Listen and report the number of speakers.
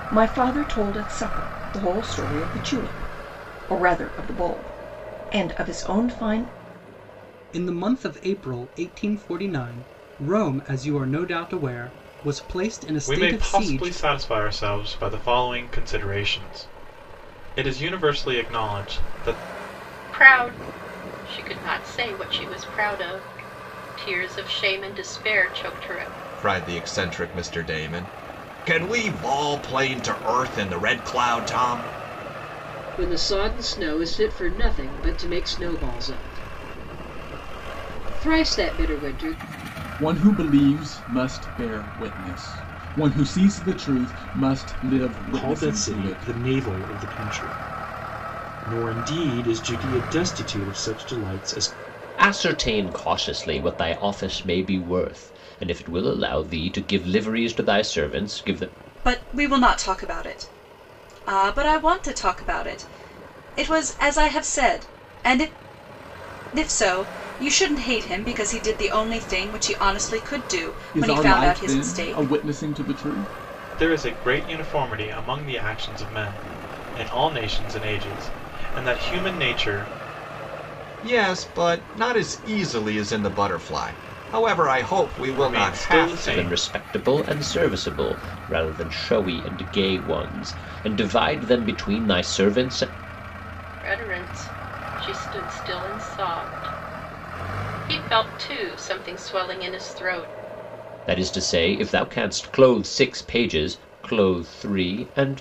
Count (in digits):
10